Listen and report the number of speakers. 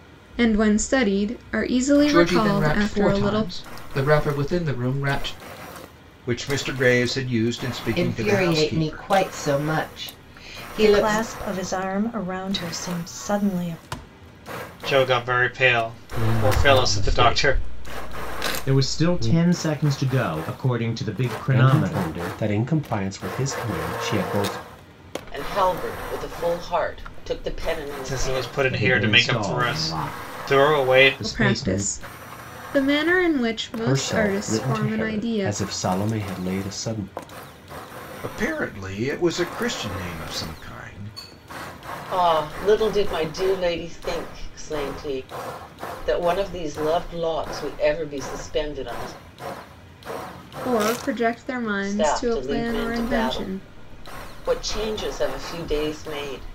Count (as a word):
ten